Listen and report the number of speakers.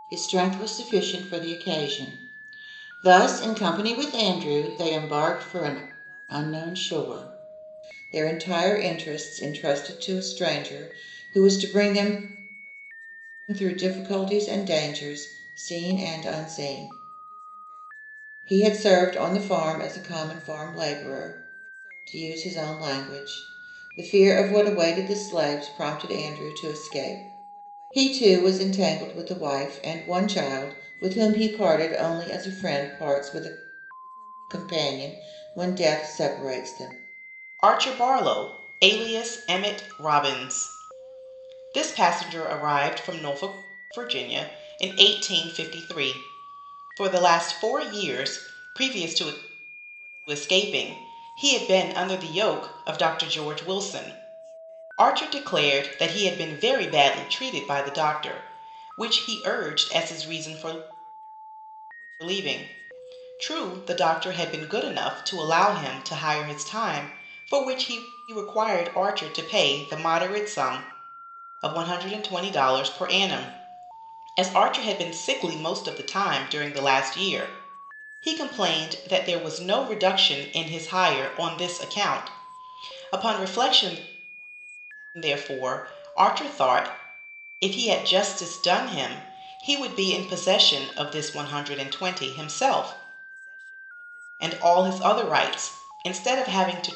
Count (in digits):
1